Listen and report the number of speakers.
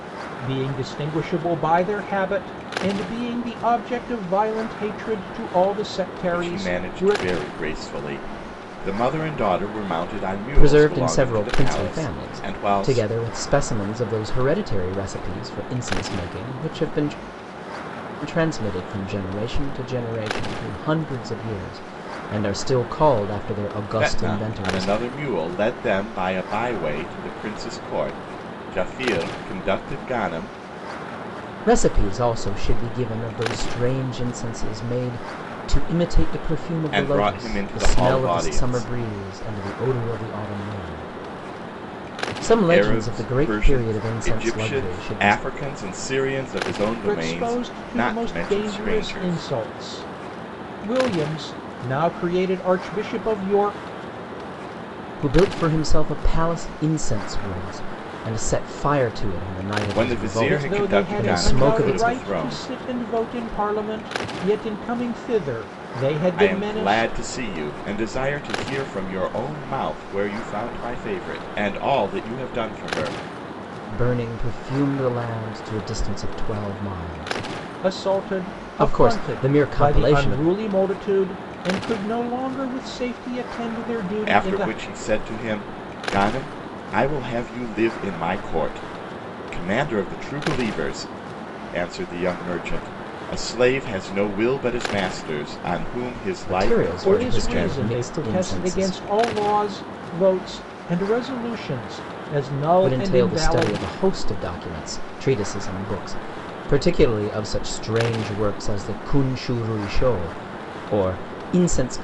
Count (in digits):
3